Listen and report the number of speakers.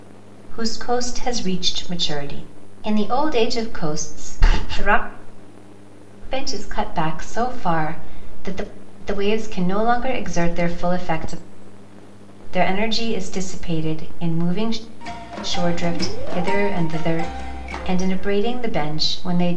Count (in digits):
1